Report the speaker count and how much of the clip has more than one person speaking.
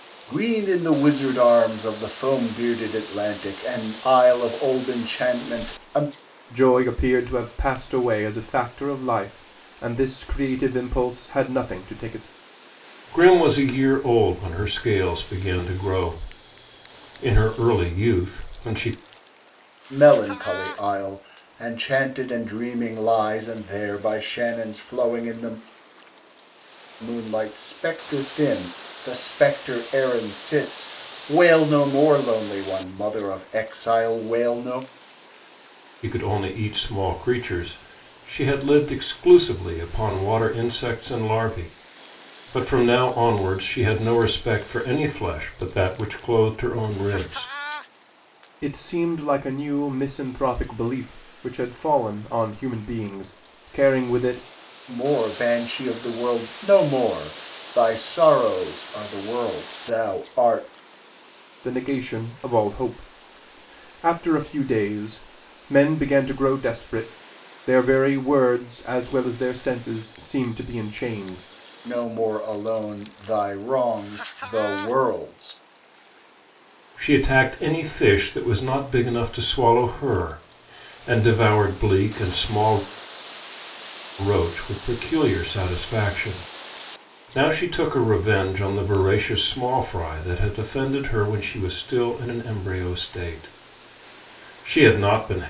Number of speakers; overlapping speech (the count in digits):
3, no overlap